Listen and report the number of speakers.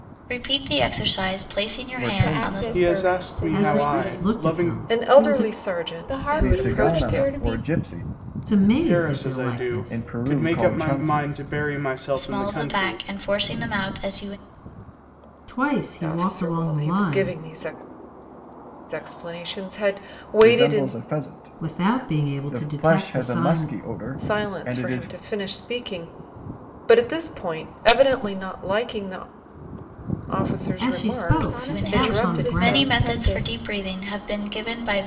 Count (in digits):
6